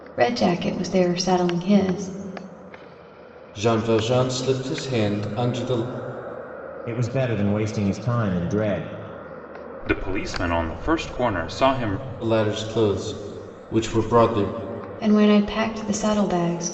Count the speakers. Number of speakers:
4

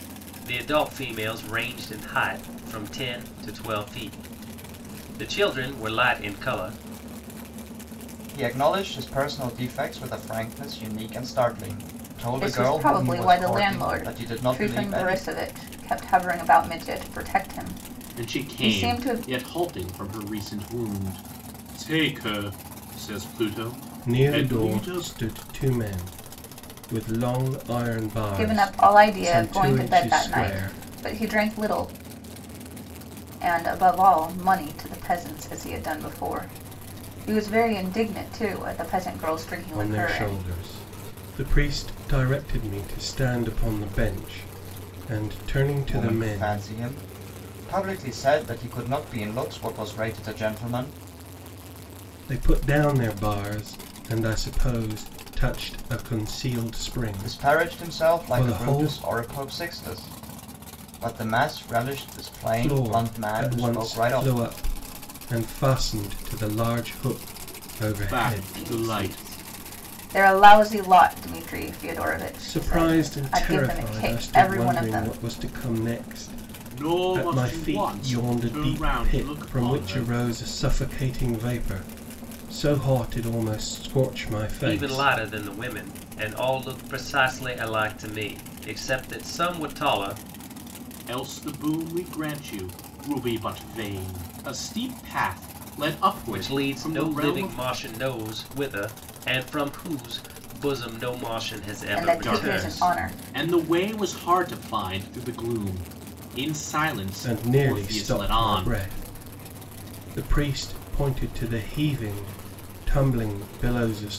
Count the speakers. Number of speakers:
5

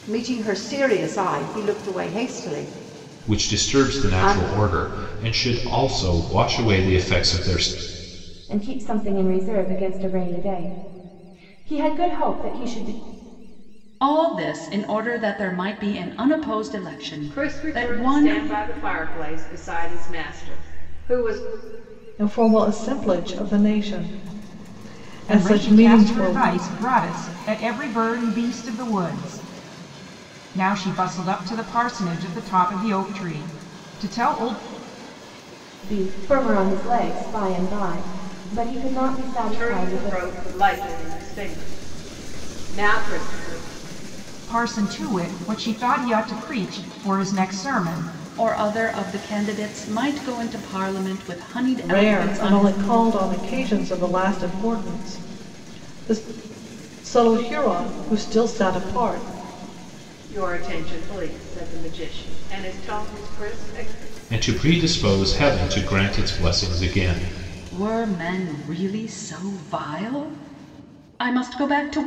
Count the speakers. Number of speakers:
7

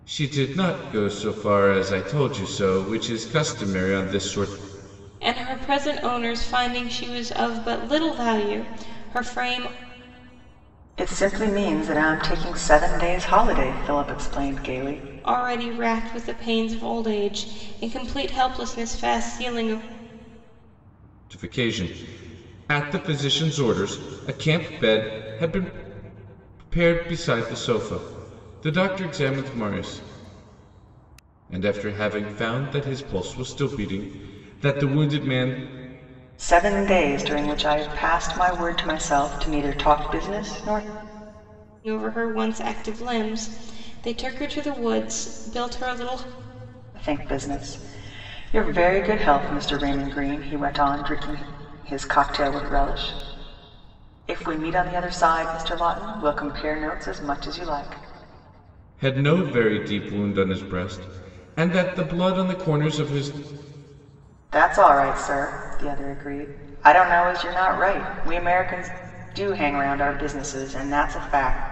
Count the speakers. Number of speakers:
3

